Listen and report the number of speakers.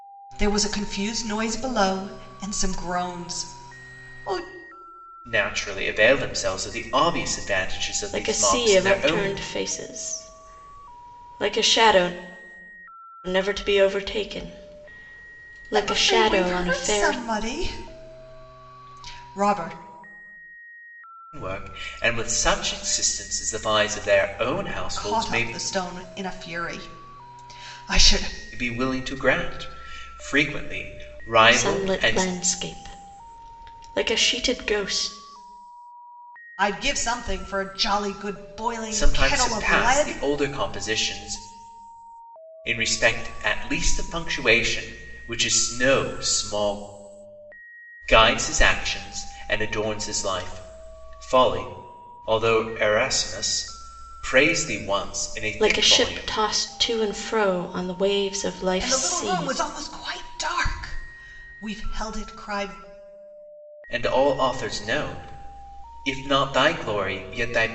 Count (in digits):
3